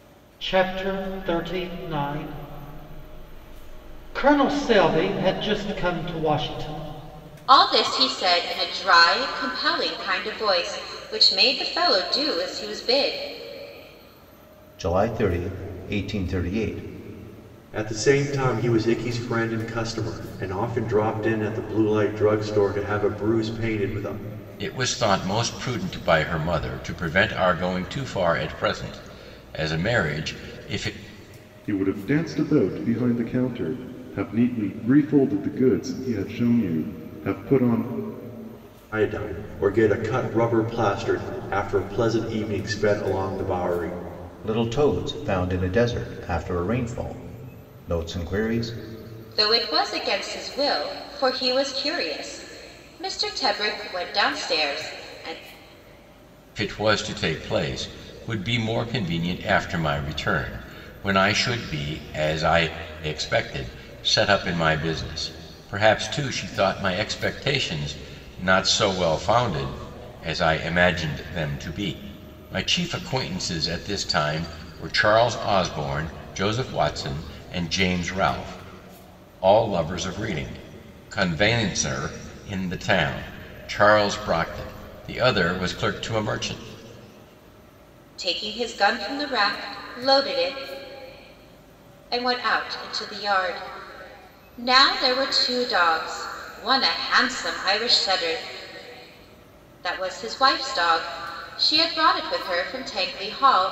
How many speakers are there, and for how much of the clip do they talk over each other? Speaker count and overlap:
six, no overlap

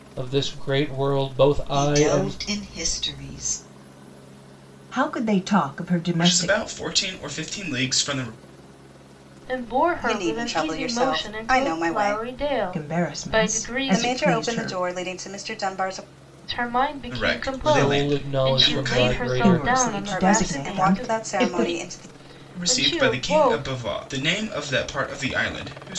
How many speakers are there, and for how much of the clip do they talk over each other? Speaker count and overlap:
six, about 45%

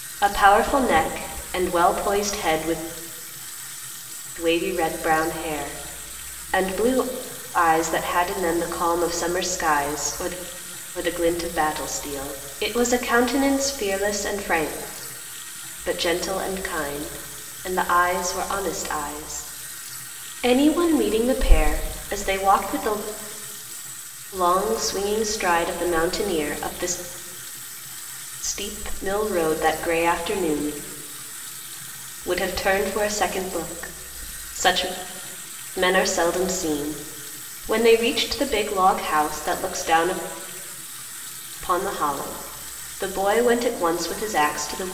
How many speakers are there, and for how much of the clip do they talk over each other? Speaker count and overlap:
one, no overlap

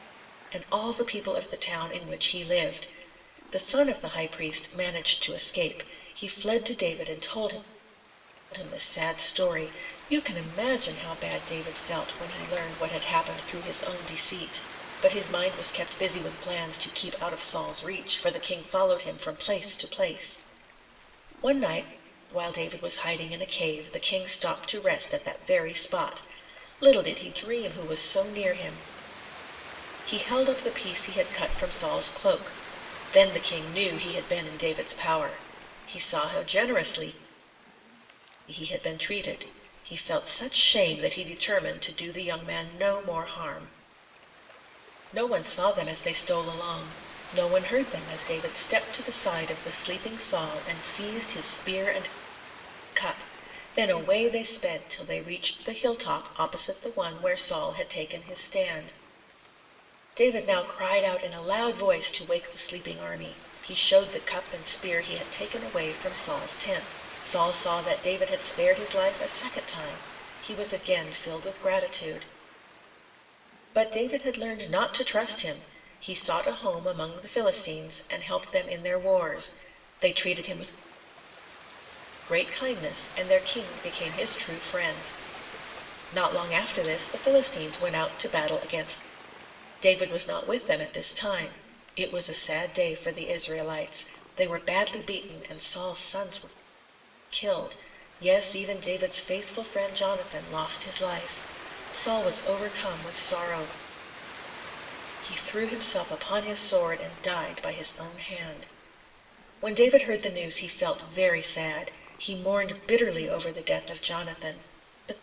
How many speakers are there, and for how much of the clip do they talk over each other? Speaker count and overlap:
one, no overlap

